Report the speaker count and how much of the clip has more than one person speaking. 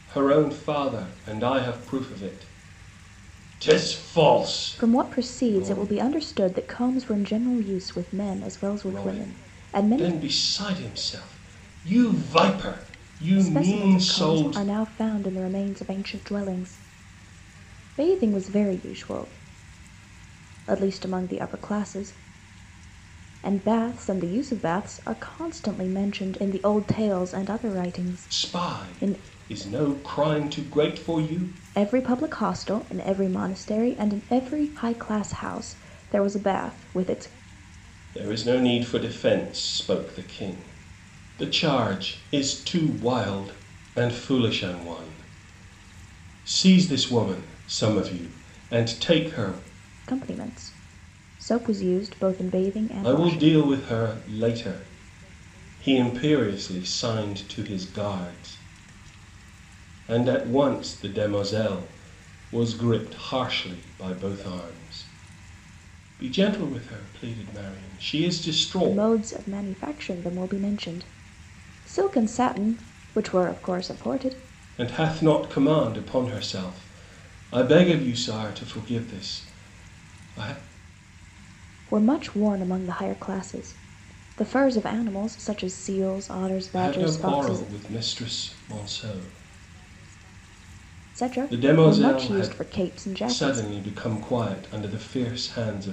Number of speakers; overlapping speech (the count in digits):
2, about 9%